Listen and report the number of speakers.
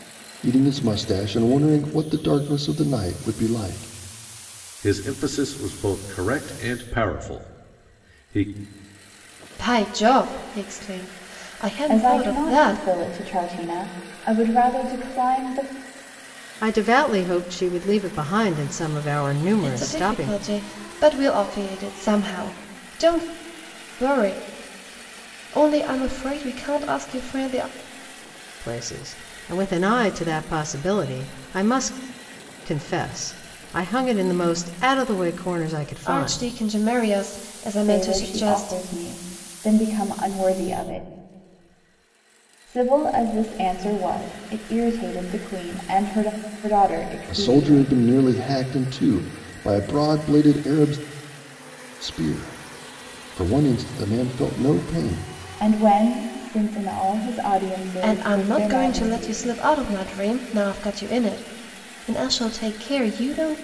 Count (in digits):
5